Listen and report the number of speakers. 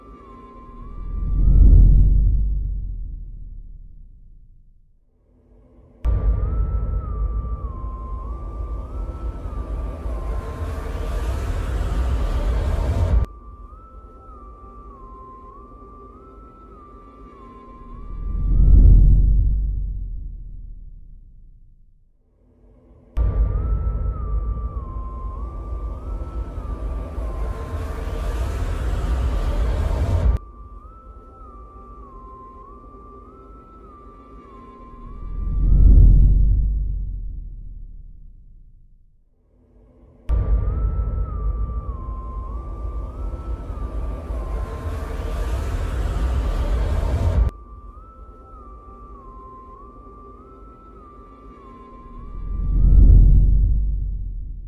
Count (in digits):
0